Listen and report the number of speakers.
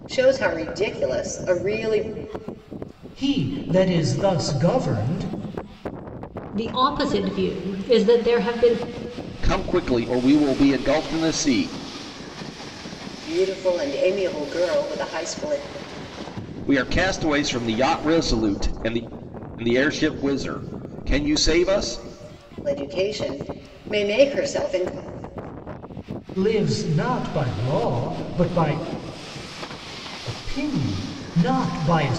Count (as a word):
four